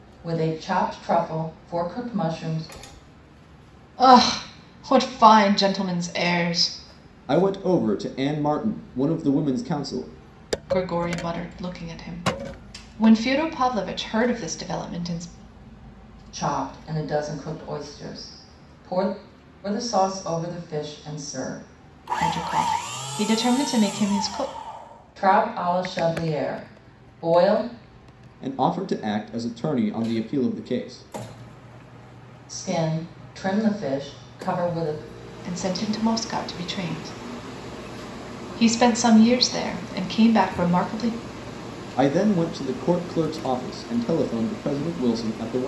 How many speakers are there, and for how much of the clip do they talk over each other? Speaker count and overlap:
3, no overlap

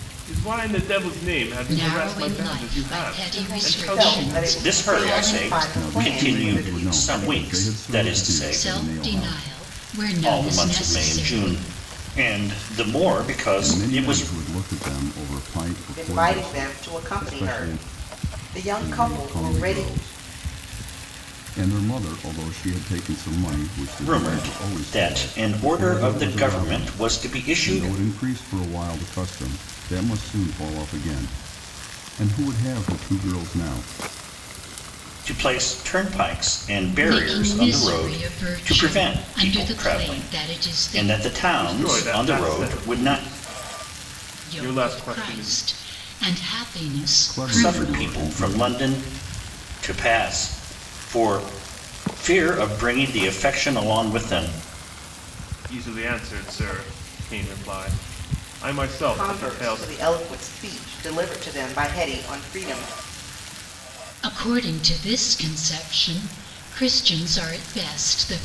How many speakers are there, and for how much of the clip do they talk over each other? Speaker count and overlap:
5, about 38%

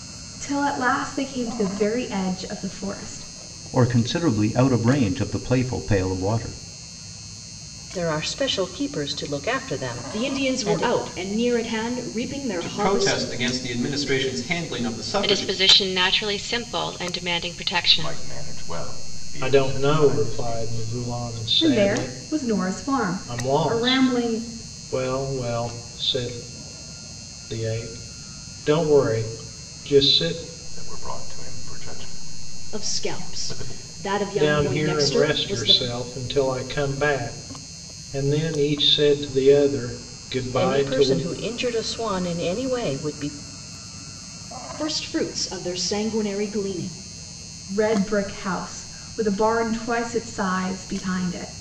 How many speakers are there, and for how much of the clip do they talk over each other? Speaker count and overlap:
8, about 17%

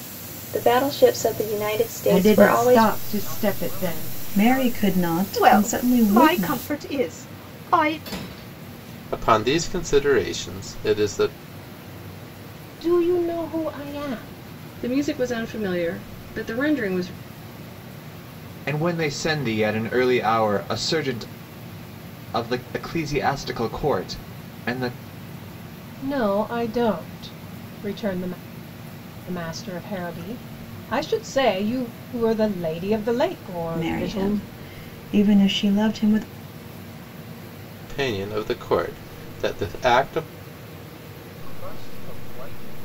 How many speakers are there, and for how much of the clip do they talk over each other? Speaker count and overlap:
9, about 12%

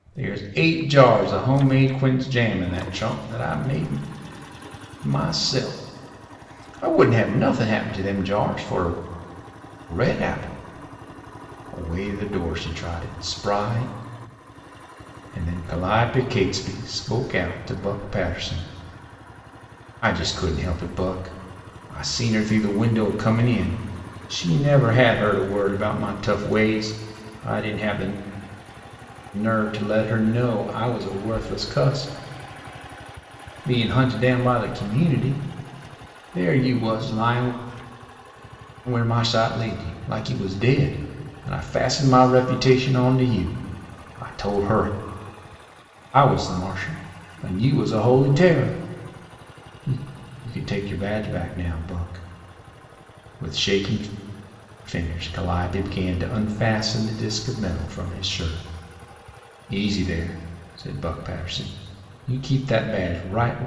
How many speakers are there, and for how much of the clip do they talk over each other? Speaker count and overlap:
1, no overlap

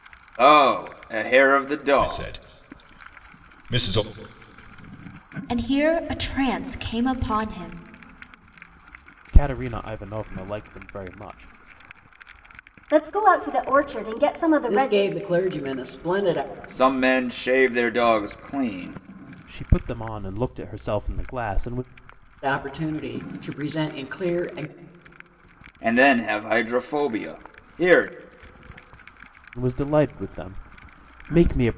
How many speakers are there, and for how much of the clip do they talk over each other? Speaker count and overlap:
6, about 2%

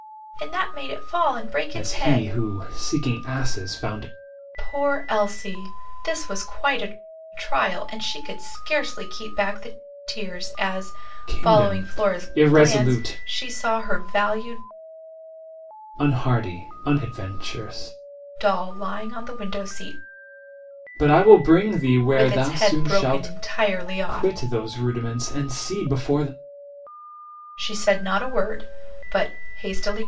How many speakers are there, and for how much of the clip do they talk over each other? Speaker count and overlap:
2, about 13%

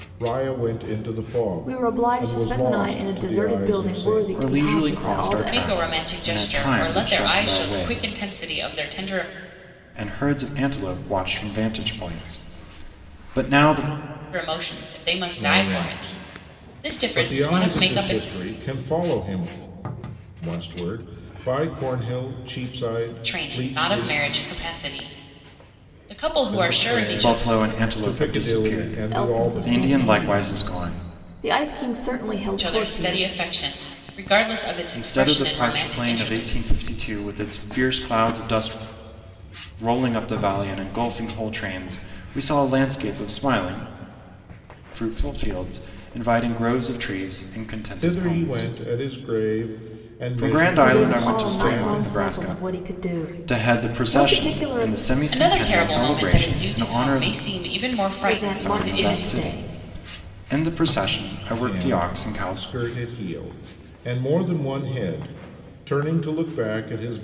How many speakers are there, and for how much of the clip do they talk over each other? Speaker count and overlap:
4, about 40%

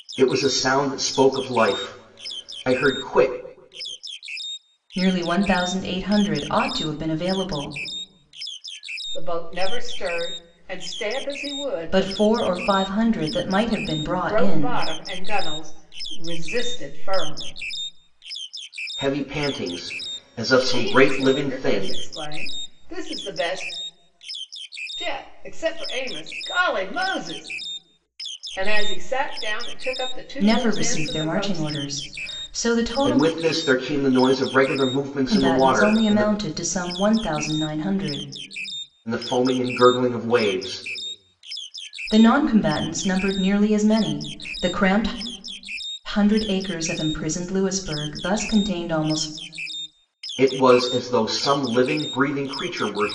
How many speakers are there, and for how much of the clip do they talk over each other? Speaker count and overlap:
3, about 9%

